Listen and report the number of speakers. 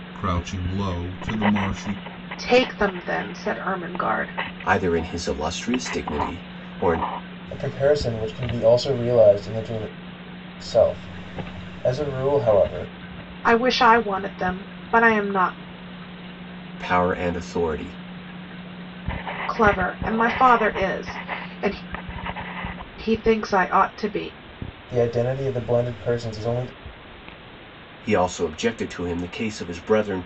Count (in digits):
4